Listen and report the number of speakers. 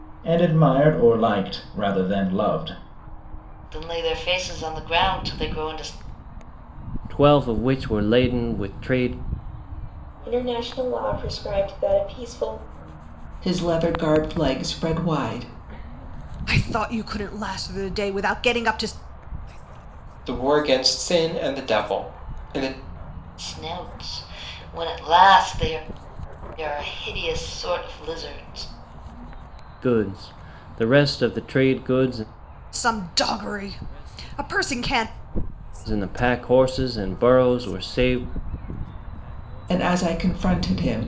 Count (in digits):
7